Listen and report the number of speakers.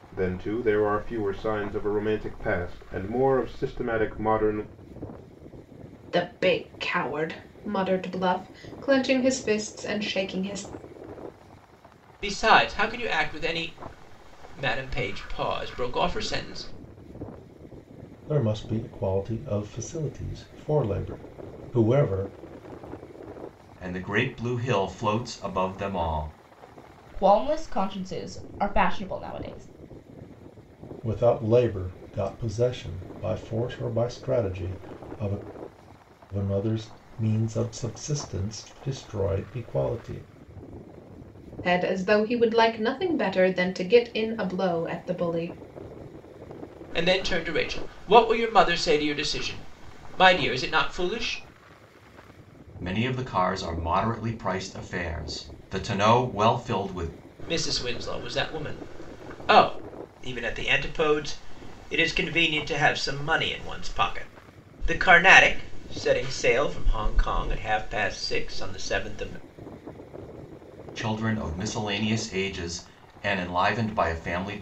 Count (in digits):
6